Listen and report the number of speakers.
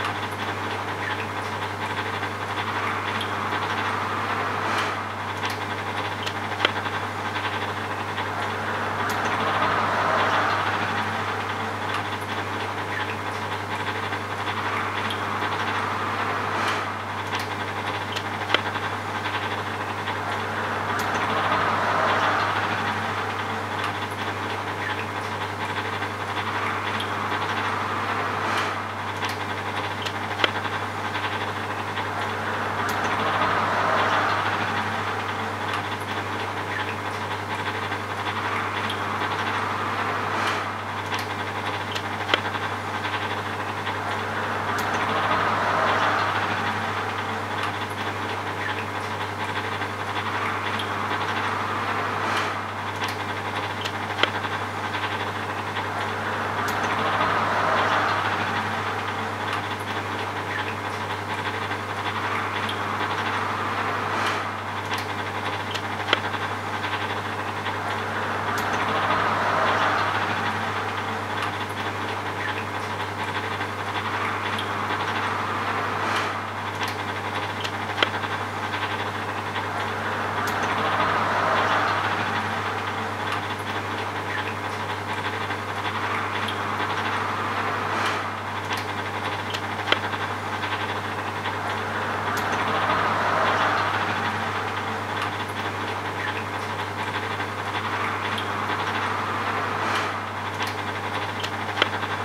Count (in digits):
0